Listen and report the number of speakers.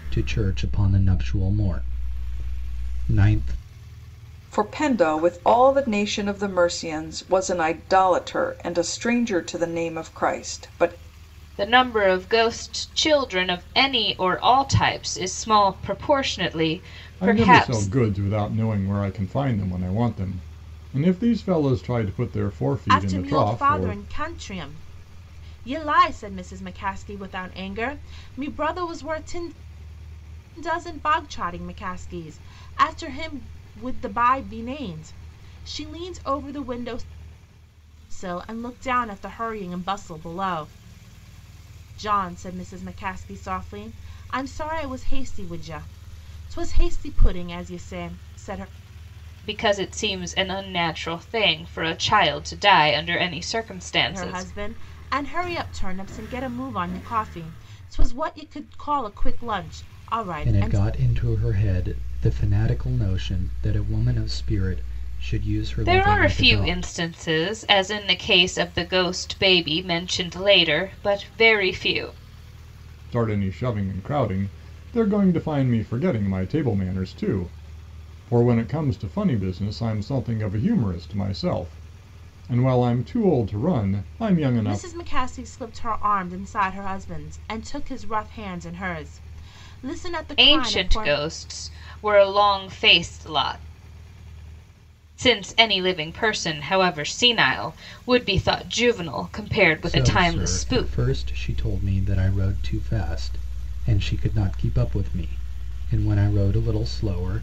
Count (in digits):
5